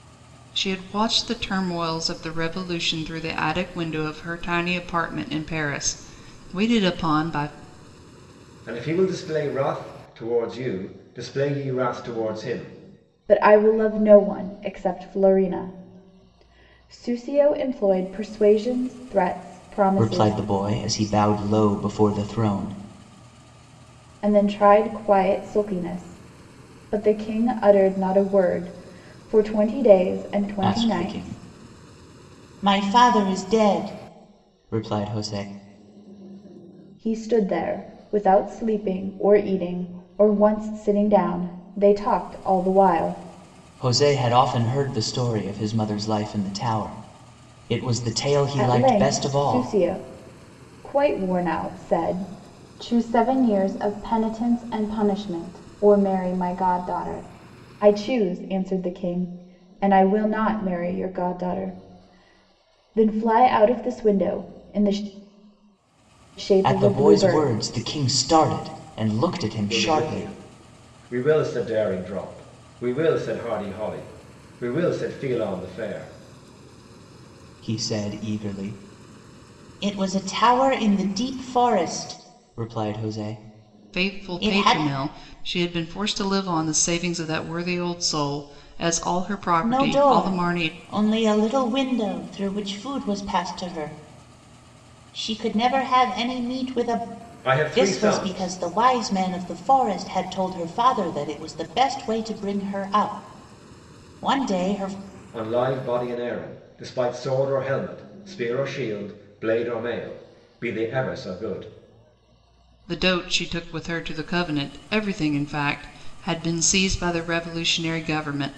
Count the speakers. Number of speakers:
4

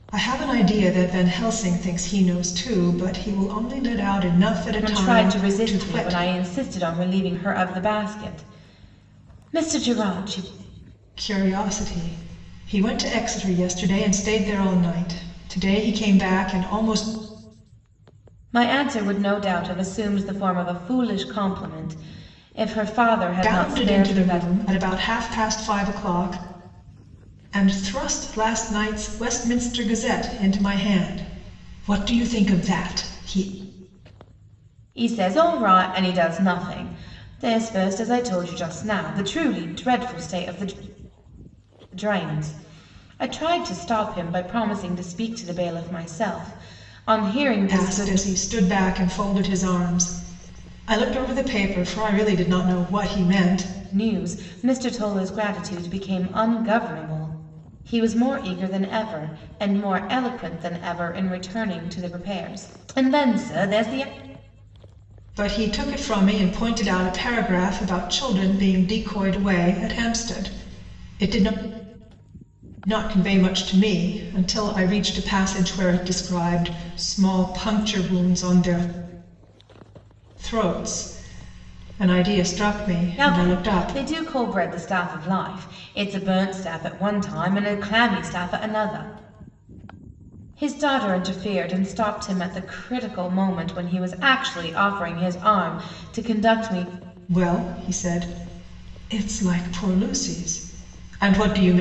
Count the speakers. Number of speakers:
2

